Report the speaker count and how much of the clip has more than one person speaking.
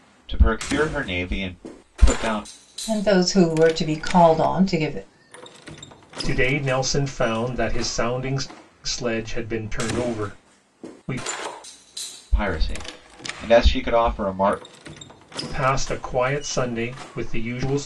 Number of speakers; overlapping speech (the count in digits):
3, no overlap